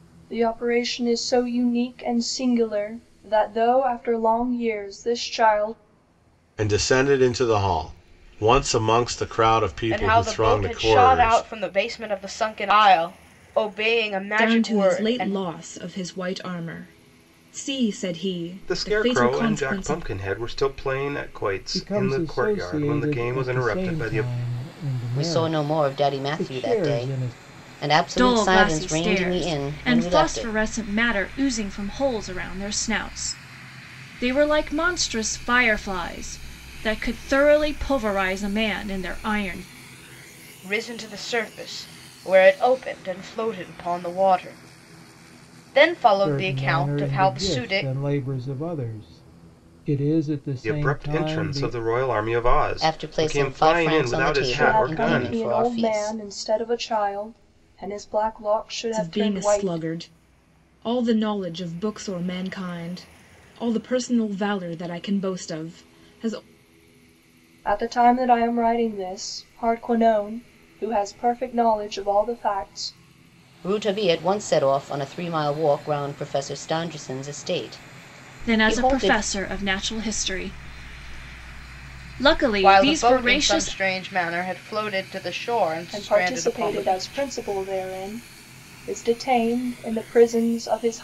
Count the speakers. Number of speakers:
eight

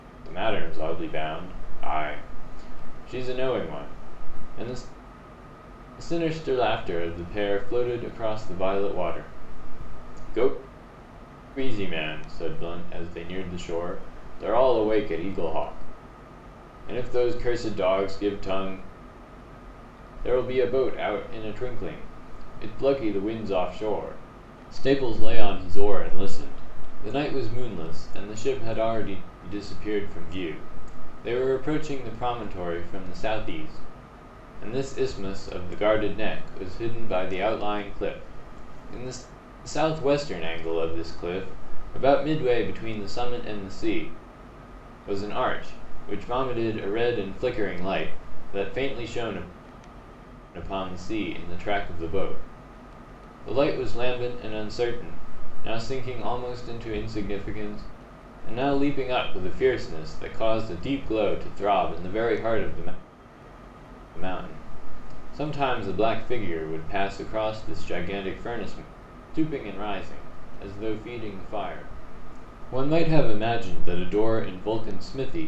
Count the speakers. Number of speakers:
one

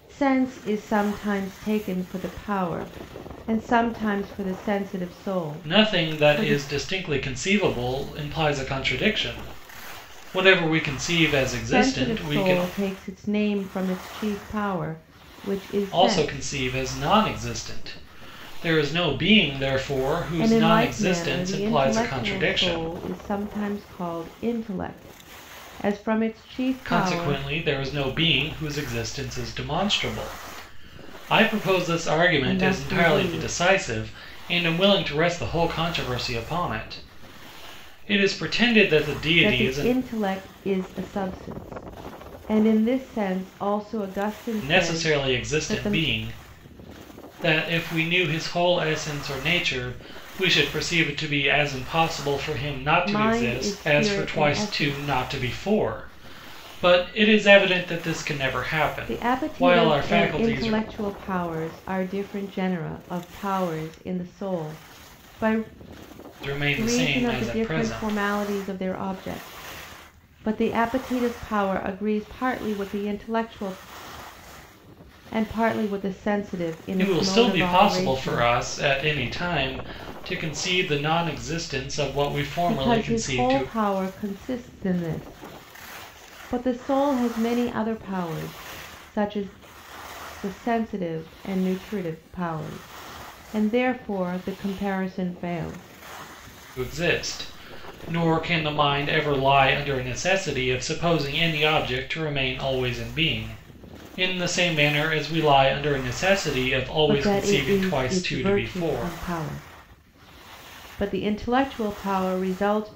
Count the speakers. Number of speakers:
two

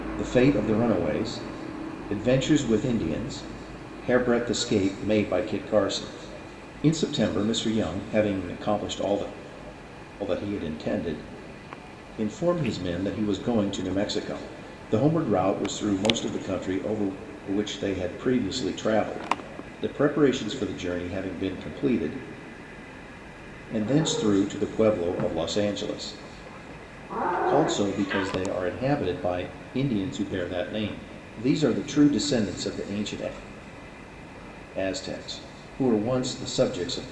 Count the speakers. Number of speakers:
one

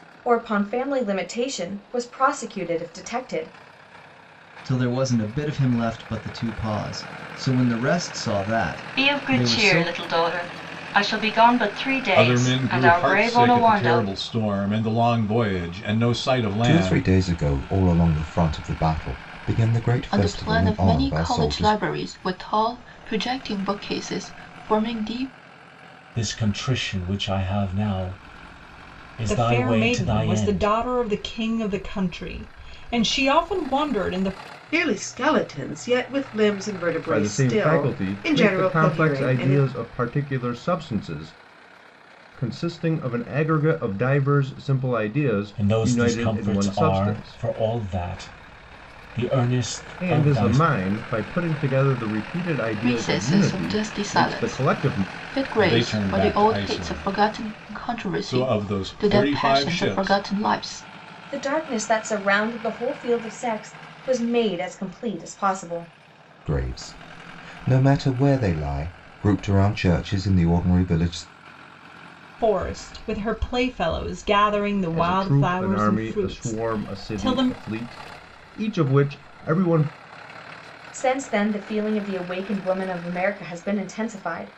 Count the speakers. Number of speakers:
ten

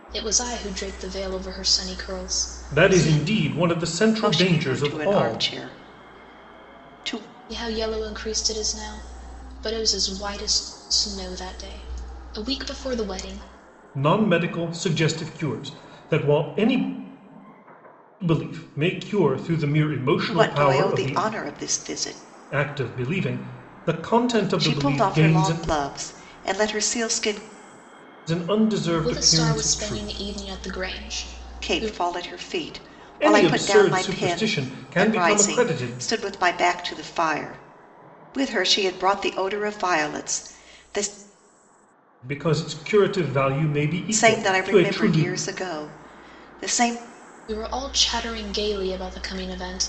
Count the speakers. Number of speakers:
three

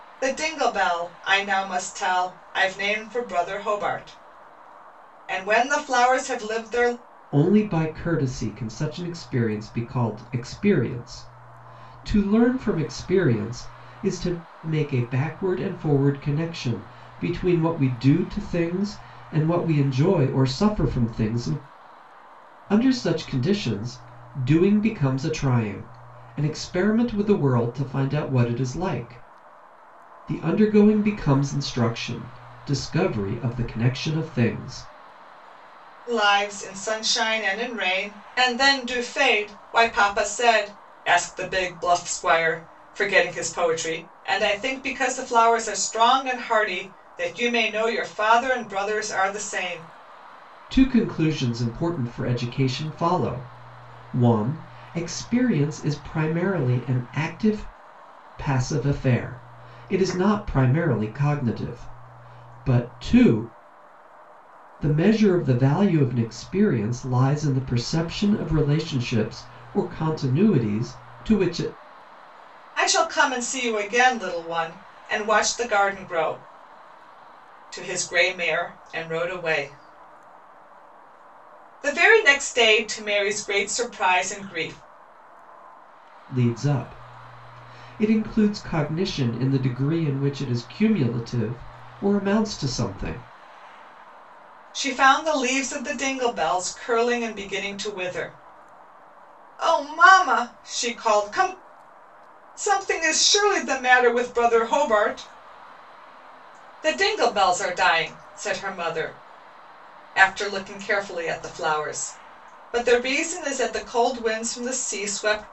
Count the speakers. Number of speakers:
two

